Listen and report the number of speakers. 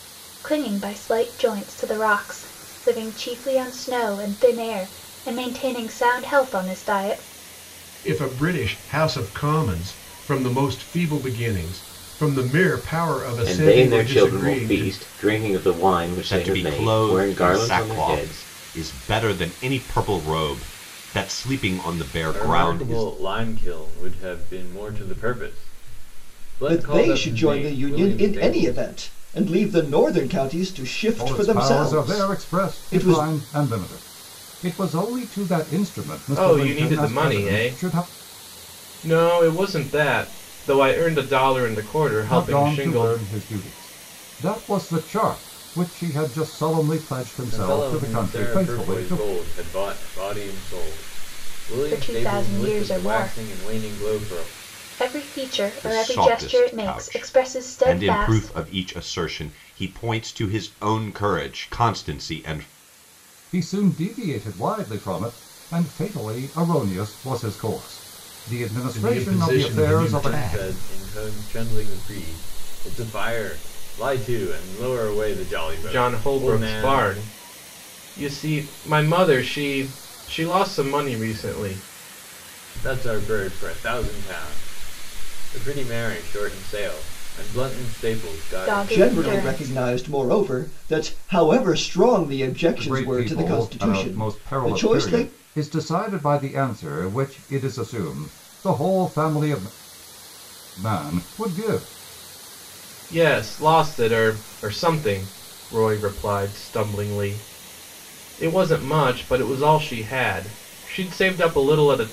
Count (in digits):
8